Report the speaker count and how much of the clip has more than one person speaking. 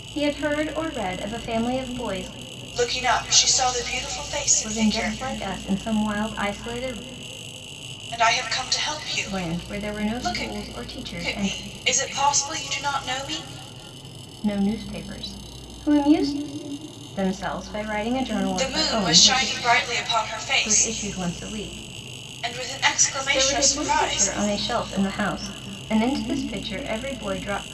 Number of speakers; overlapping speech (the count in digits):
2, about 17%